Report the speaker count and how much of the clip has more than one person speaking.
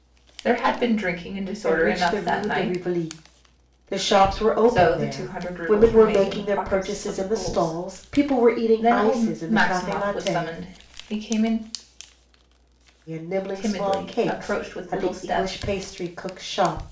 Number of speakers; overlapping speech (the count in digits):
2, about 52%